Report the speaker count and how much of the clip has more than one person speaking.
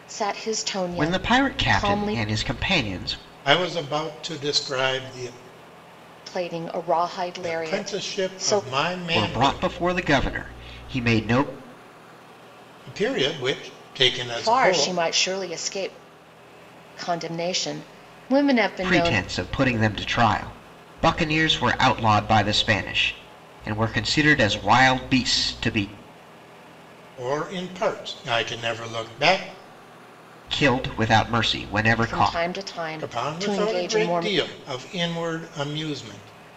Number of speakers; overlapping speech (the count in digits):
3, about 17%